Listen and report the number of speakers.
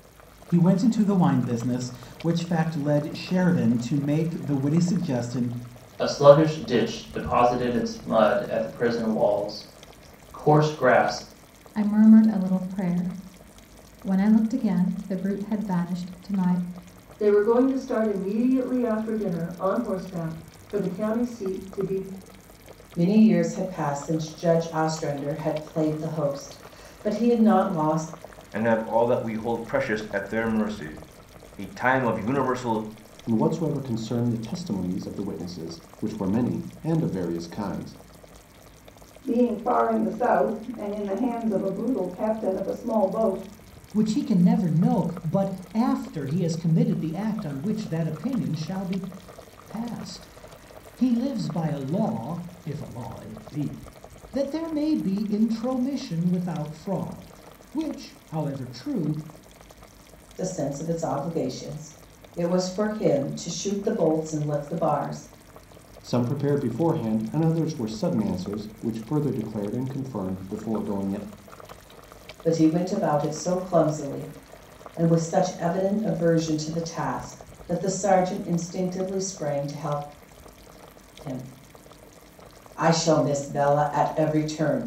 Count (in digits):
9